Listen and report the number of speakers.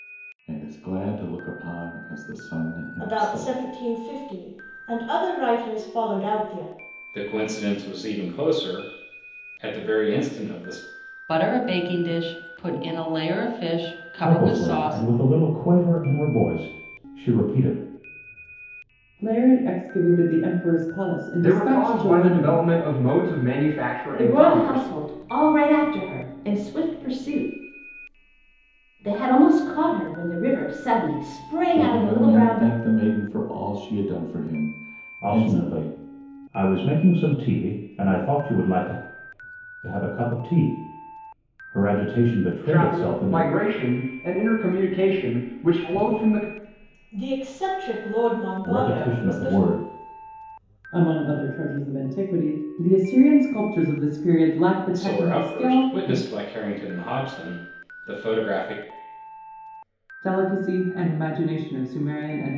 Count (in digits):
8